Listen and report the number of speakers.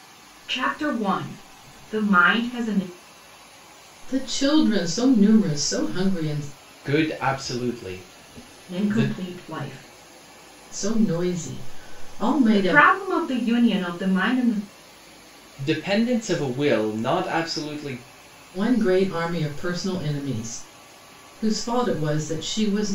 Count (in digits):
3